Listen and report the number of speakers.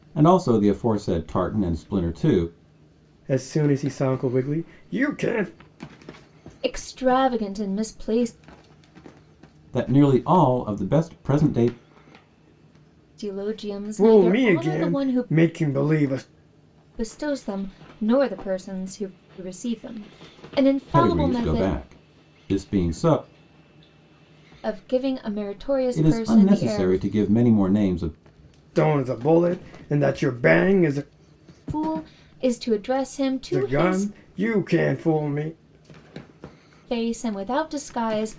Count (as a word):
three